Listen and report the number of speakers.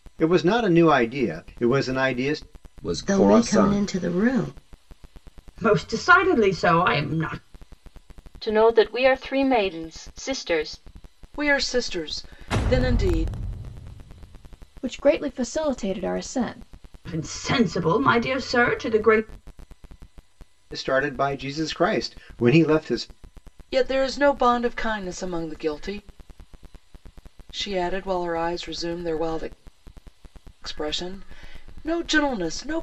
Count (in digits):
7